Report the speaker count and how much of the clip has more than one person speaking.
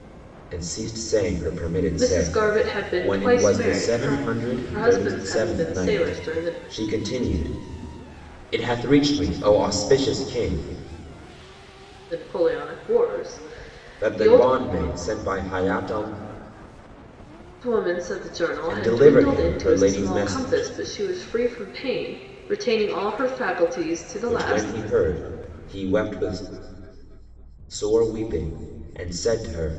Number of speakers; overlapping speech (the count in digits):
2, about 22%